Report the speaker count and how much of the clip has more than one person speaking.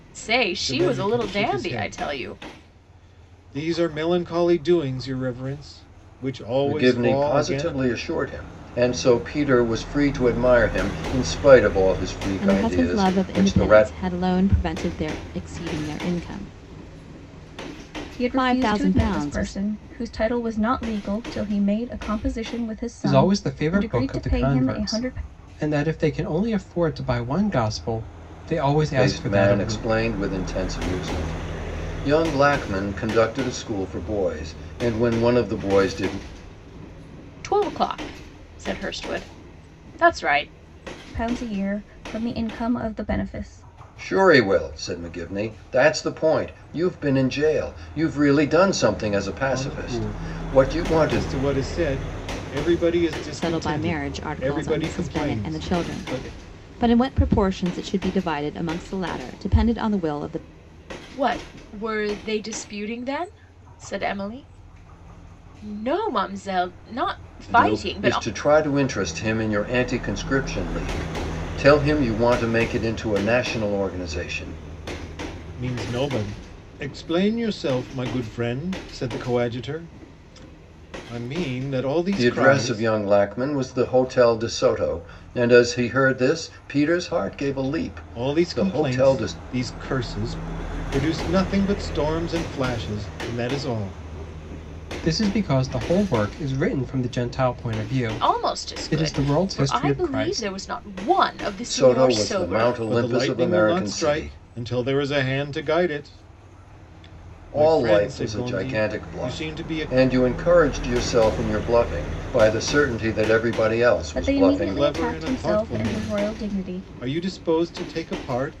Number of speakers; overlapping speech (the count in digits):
6, about 23%